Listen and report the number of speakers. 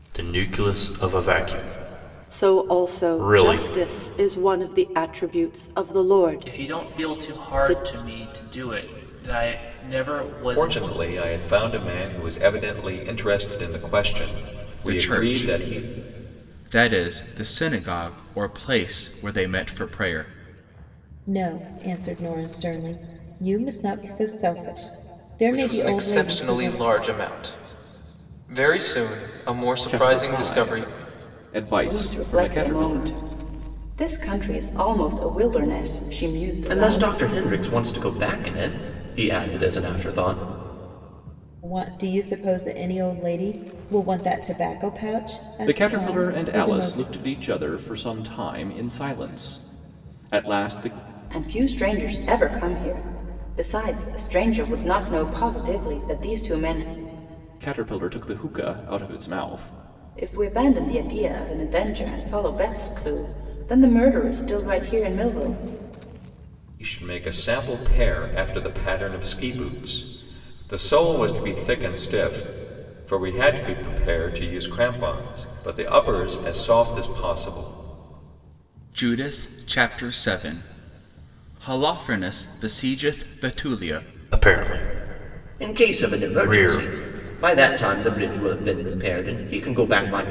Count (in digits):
10